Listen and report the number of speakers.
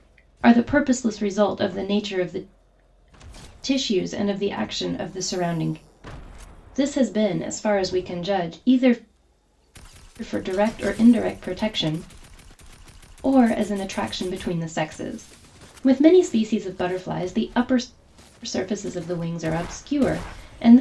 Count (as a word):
one